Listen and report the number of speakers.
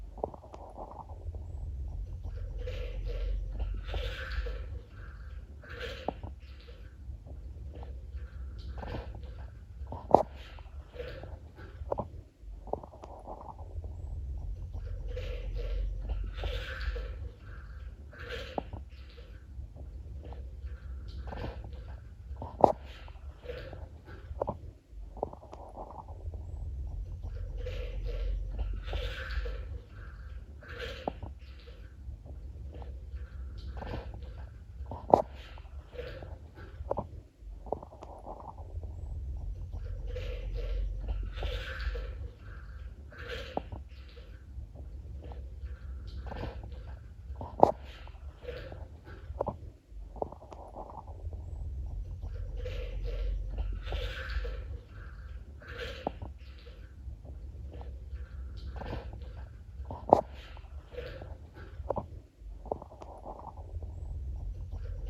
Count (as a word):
zero